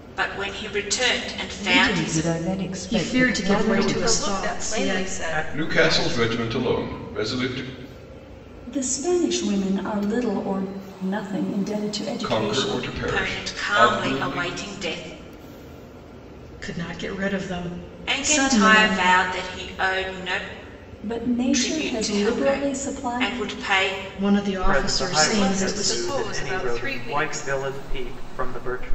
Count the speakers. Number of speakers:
seven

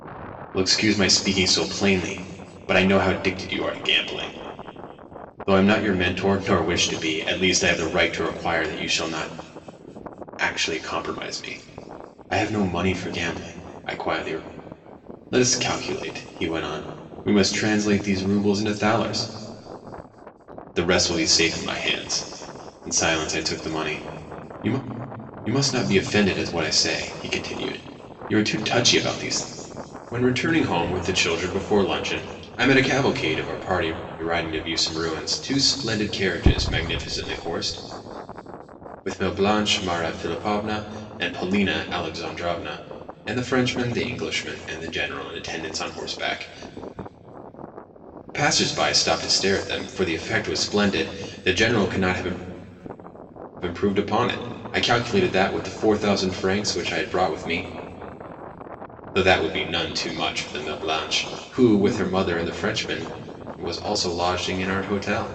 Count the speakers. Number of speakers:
one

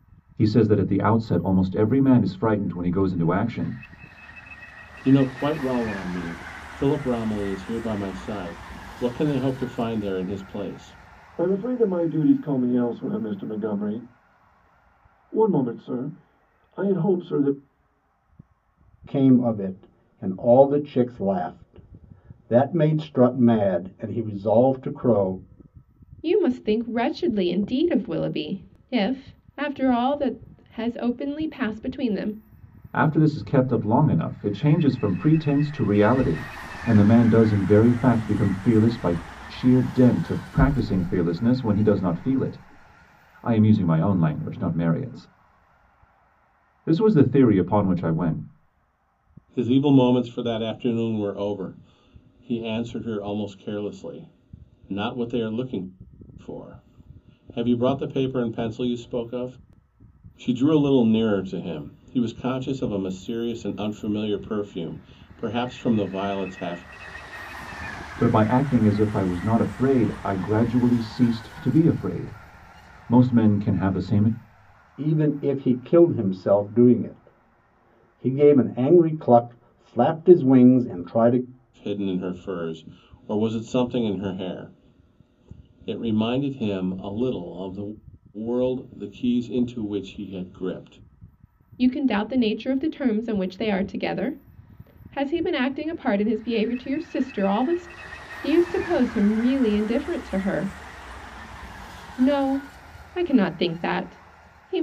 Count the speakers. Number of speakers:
five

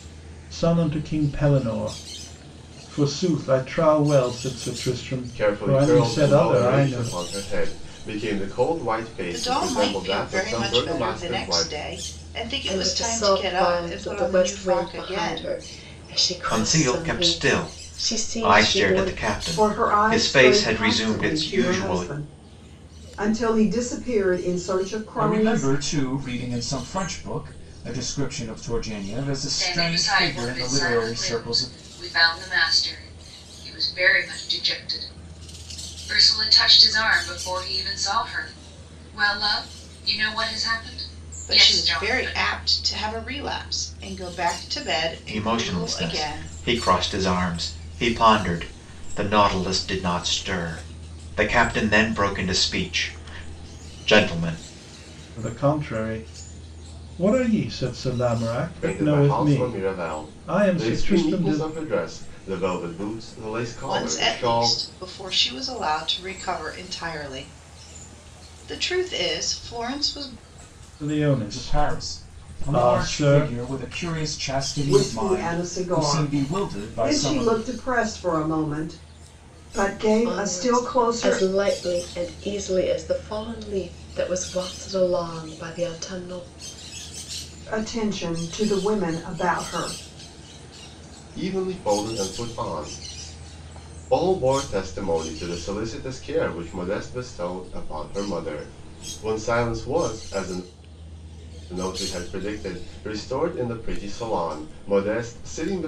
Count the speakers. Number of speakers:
eight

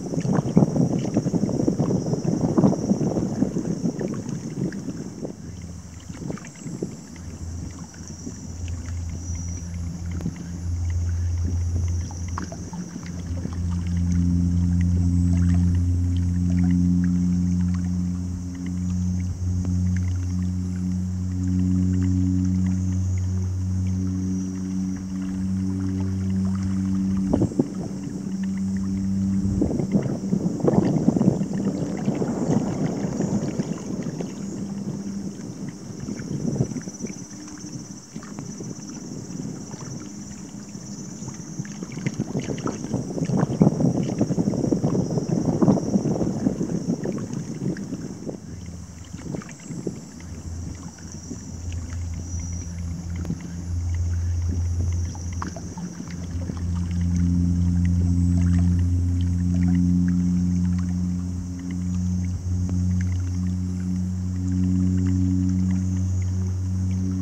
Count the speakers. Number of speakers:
zero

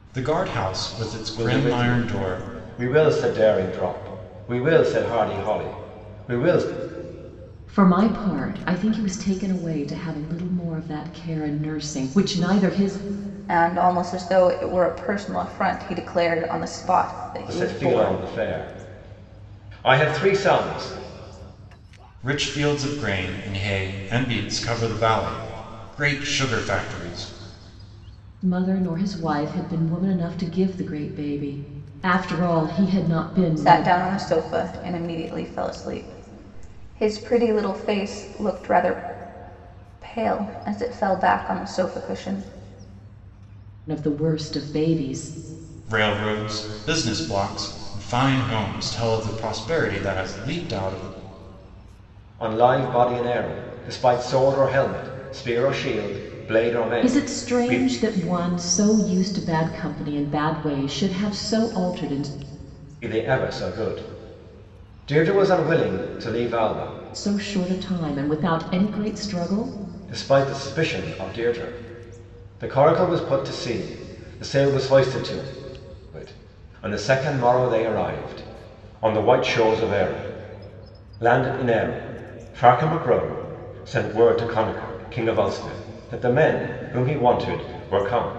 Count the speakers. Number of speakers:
four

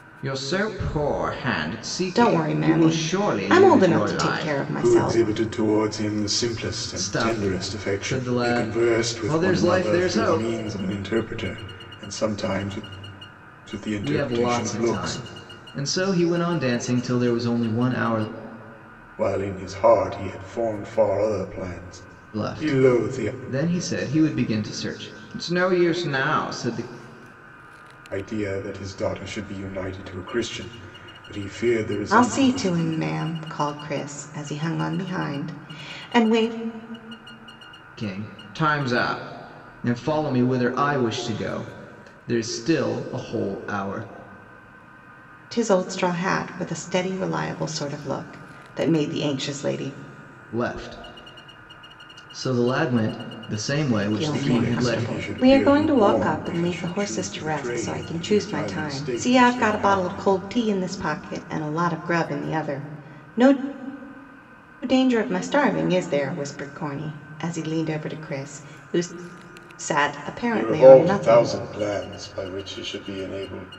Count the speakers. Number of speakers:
three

